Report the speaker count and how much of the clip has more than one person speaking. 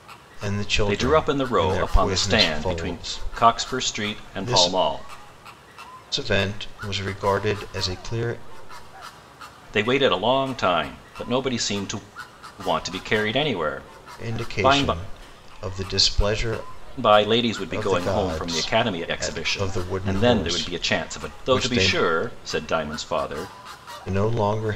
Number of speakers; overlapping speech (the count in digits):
2, about 35%